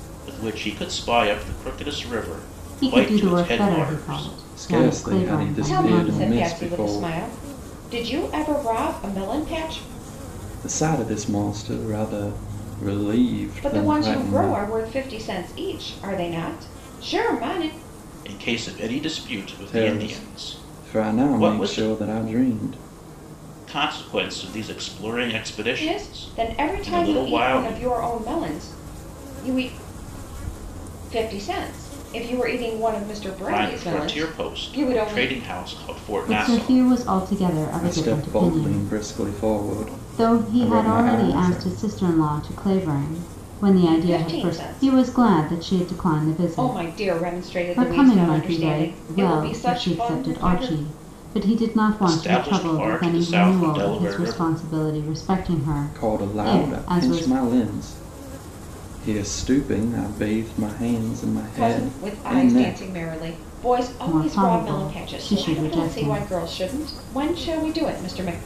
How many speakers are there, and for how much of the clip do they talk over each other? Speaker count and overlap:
four, about 42%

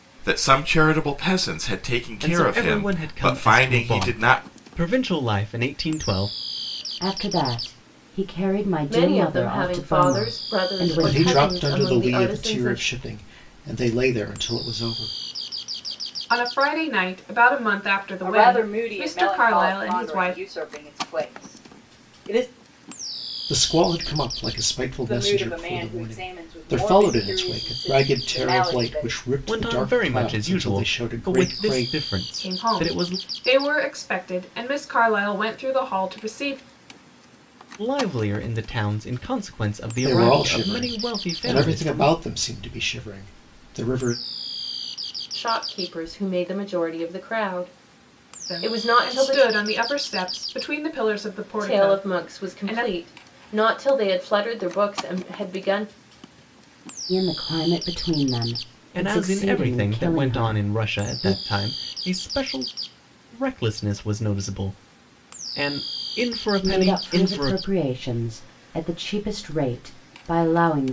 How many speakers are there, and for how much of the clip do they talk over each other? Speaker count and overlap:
seven, about 34%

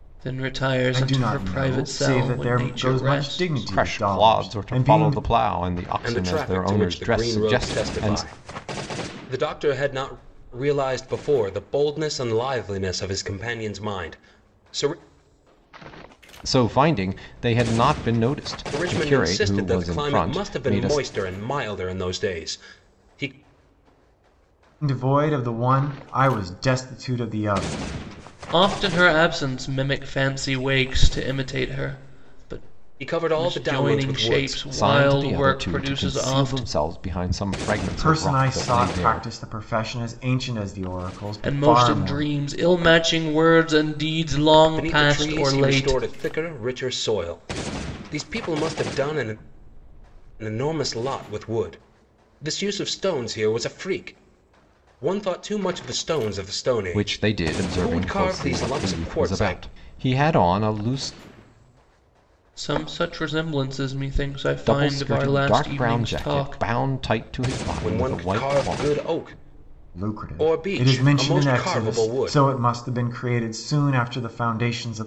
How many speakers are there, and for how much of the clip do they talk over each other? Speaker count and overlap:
four, about 32%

